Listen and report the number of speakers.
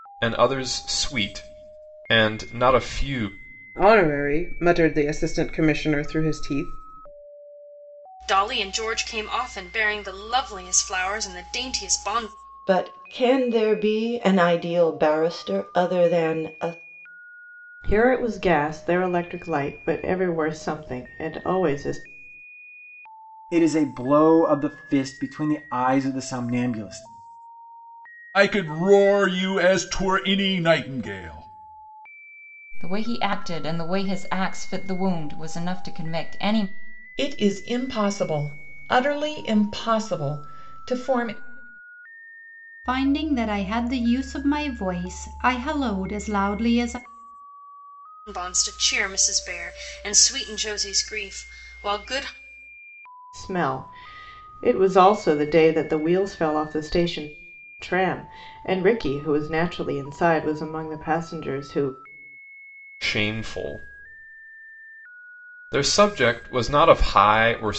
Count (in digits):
10